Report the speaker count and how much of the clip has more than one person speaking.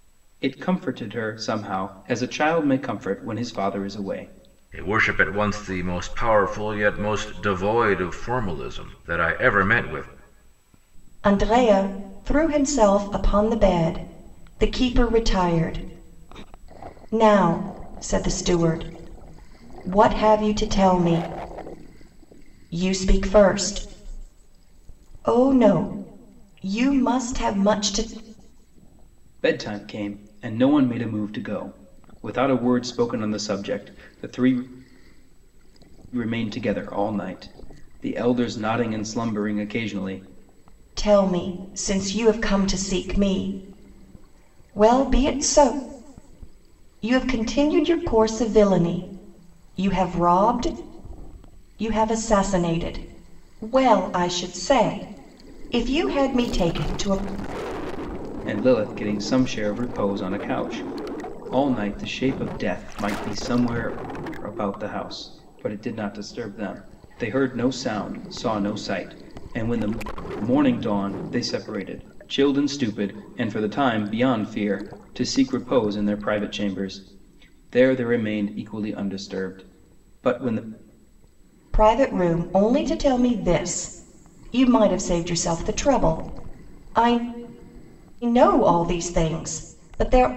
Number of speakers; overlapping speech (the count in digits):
3, no overlap